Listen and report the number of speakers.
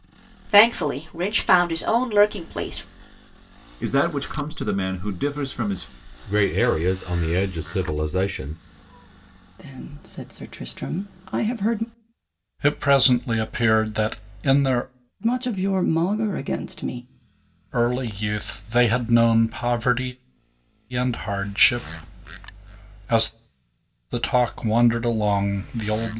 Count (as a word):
five